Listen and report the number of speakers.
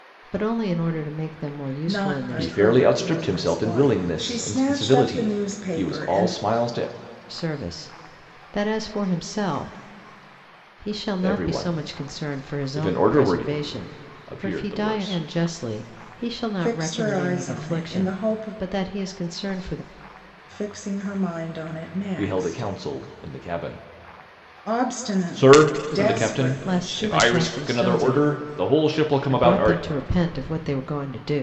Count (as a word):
three